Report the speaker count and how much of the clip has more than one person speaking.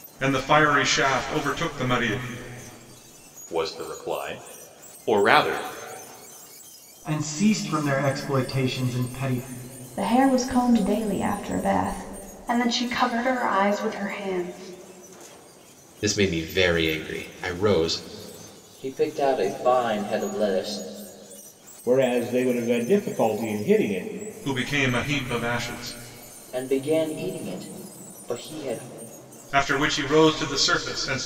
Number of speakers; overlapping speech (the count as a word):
eight, no overlap